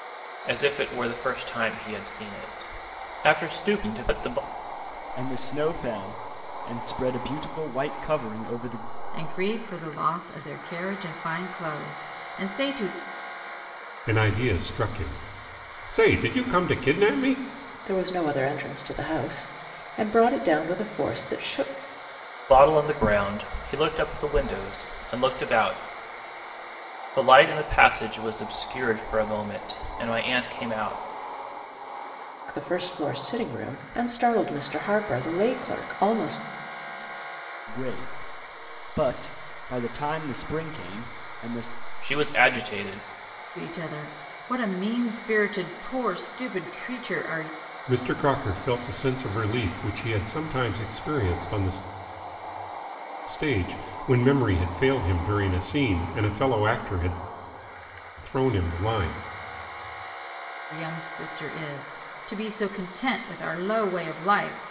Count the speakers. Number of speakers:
5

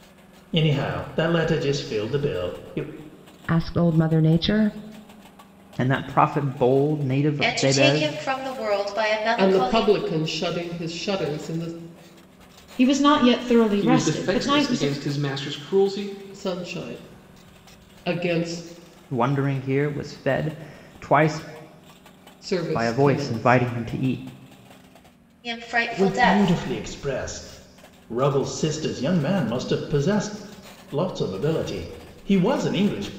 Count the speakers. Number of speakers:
7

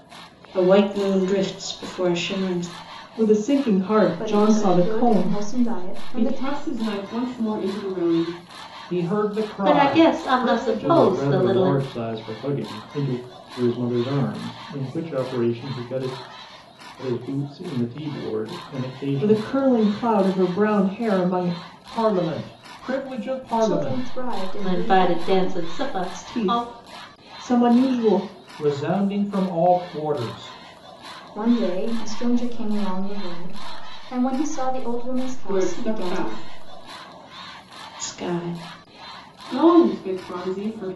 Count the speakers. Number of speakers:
7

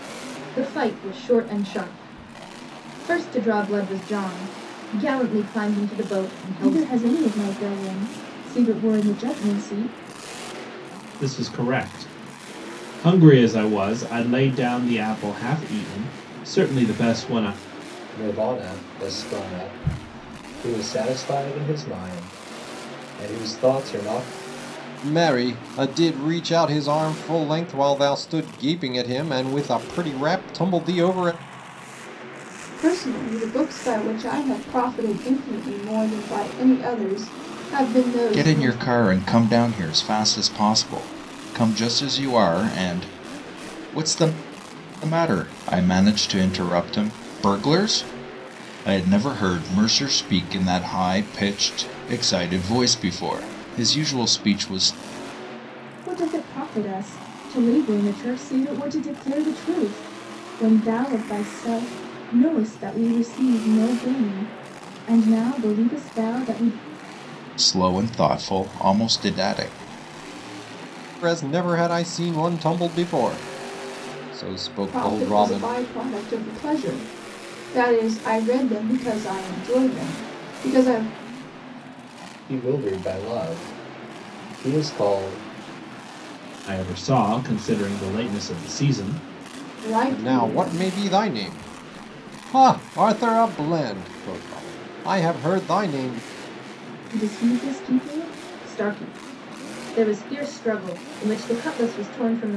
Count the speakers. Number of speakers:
7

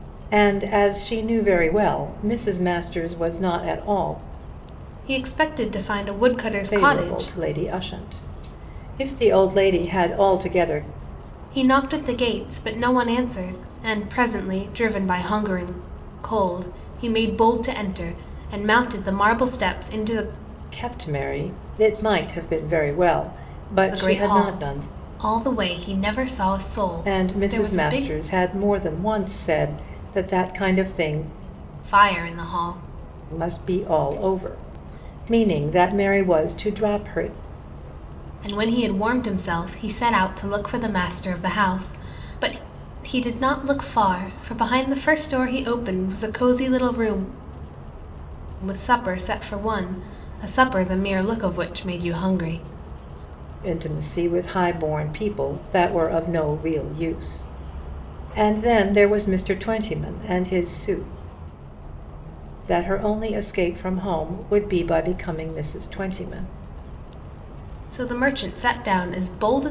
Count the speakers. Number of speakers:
2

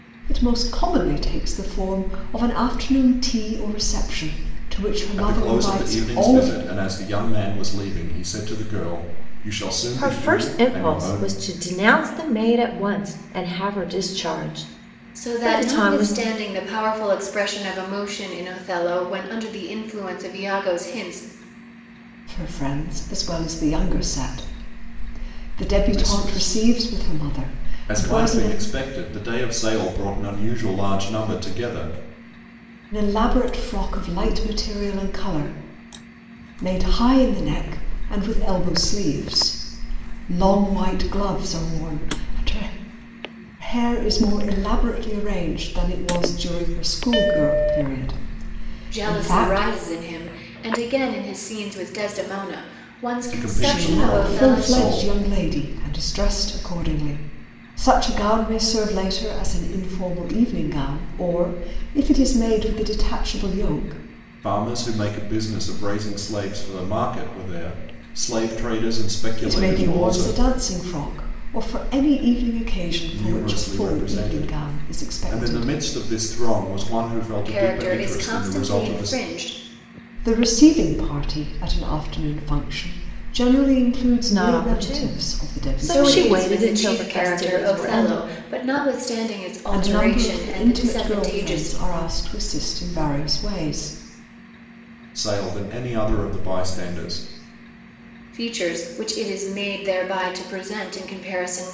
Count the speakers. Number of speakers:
4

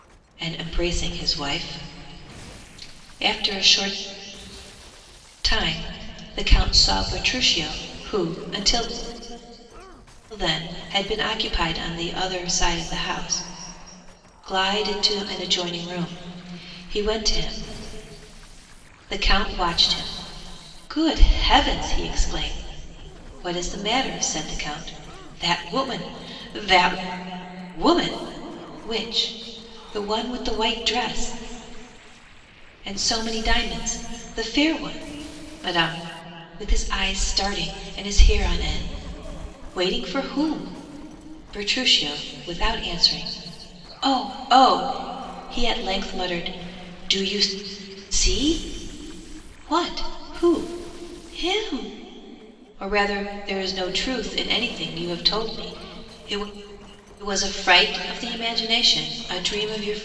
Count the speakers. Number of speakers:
1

